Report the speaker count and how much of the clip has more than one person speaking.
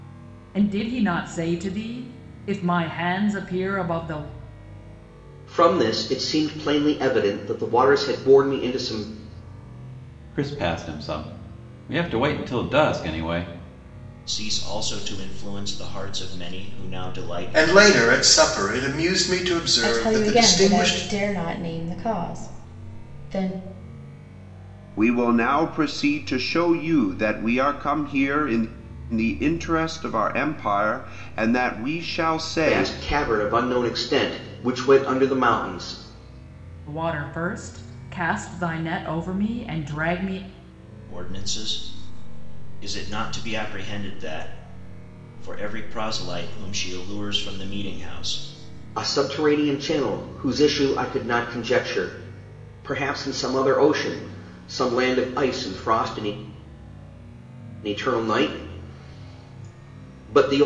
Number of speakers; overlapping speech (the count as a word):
seven, about 3%